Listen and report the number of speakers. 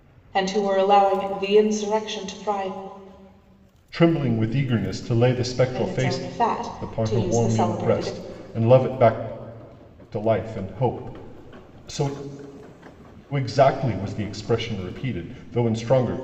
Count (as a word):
two